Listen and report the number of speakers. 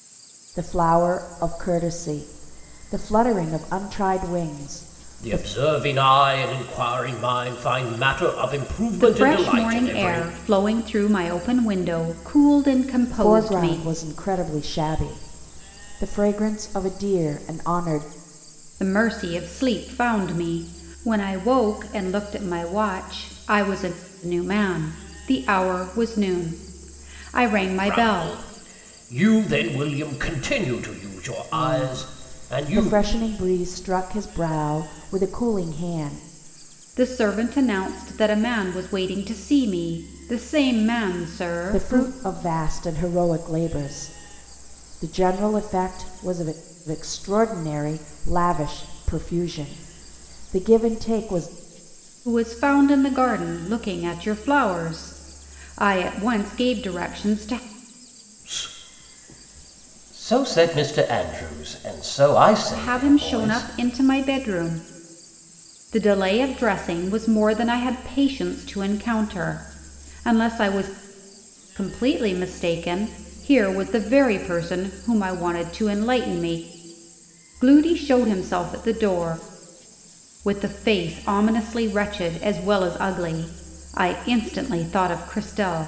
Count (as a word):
three